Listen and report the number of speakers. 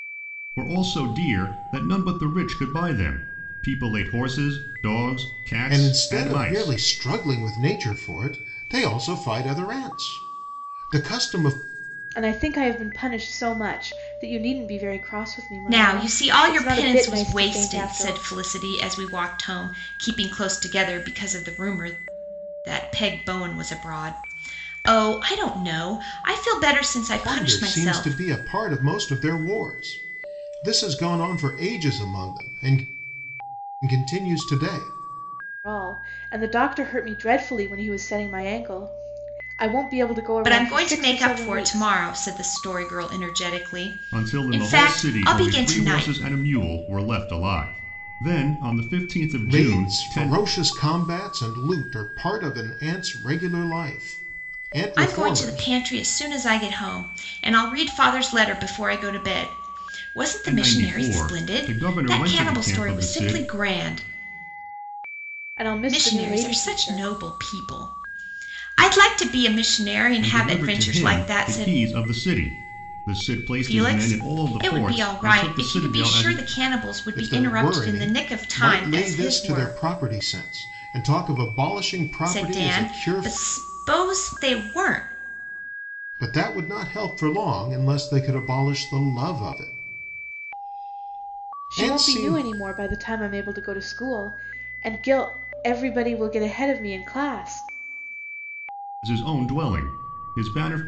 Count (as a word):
four